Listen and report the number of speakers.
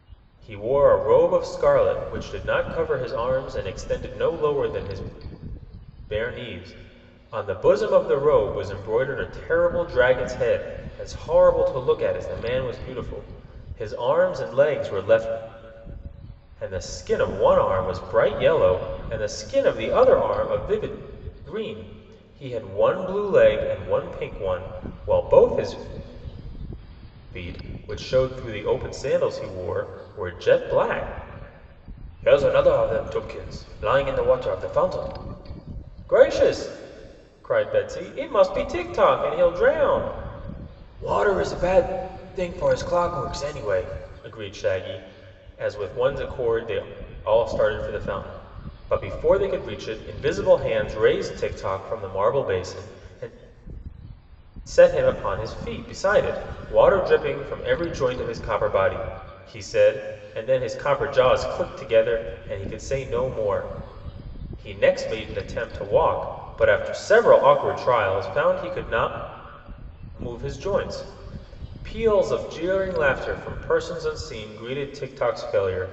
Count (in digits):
1